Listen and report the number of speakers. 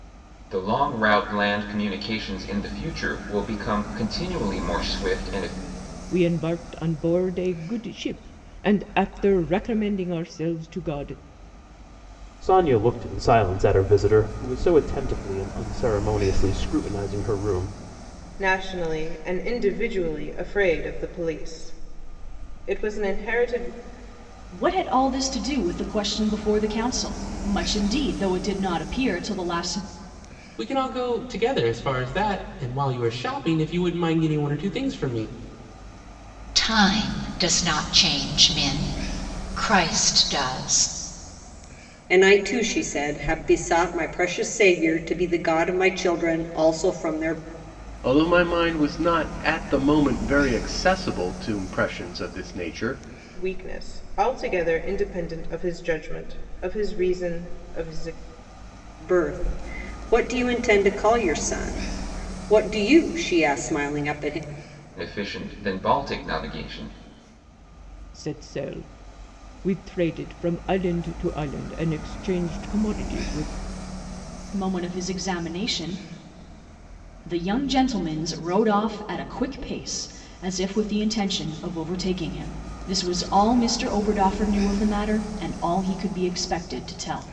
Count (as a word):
nine